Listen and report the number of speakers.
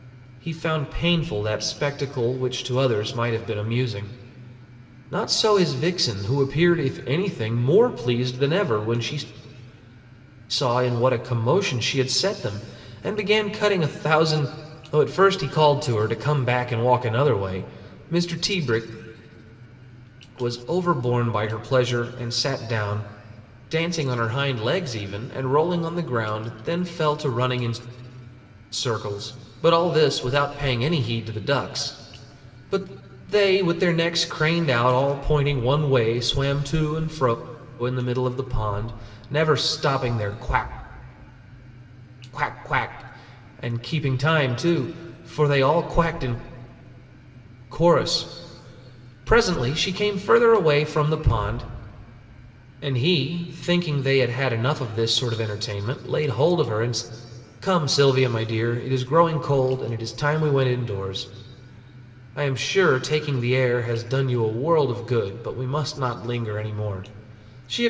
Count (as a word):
one